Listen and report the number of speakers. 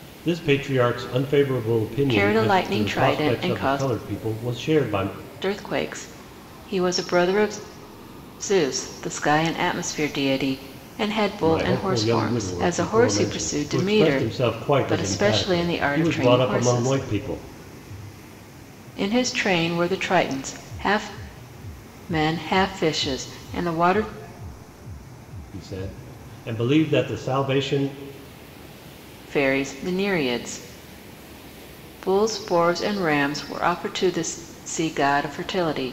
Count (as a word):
two